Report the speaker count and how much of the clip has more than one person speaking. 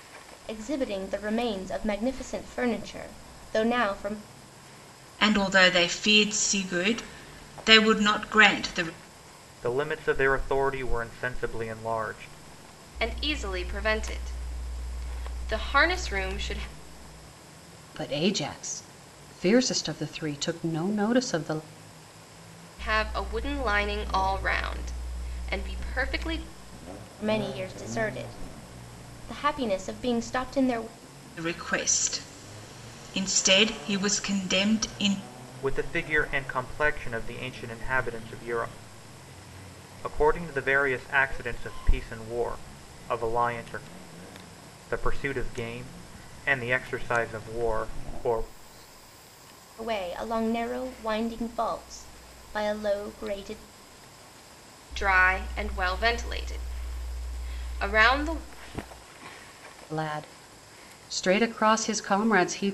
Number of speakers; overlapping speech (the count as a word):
five, no overlap